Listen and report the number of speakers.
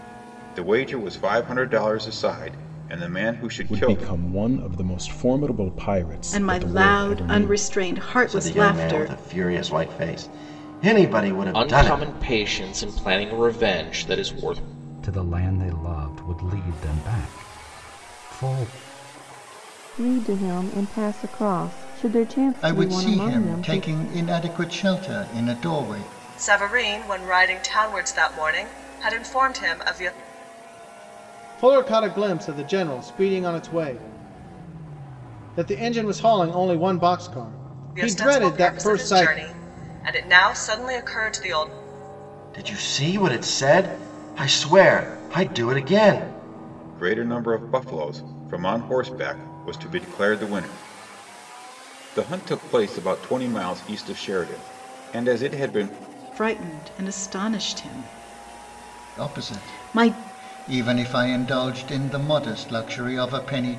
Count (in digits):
10